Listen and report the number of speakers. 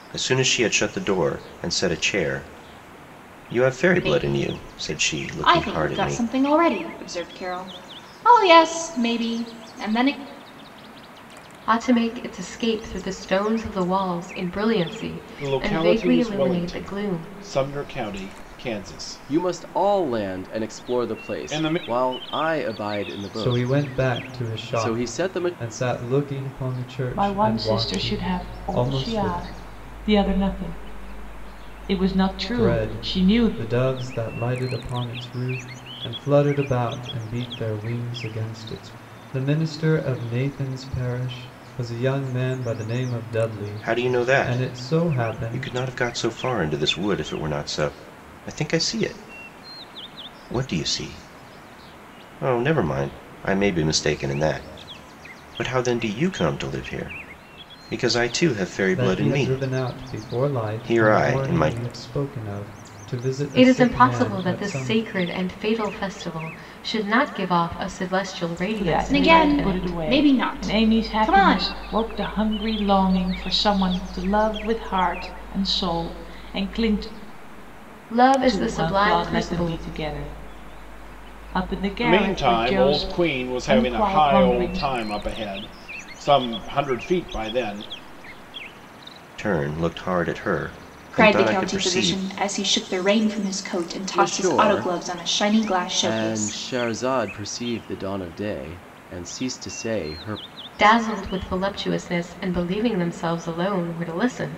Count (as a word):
seven